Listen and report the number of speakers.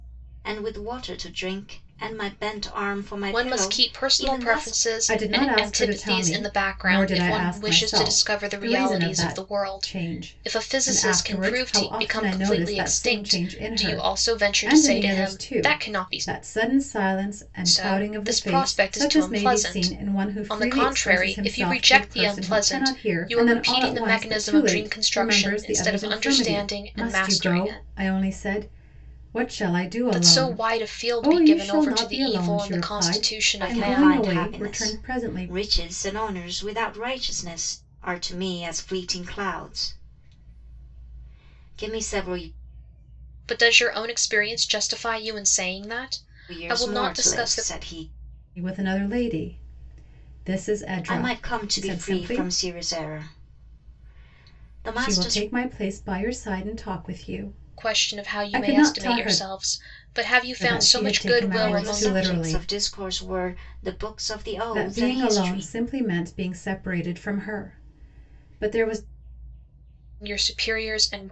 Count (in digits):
3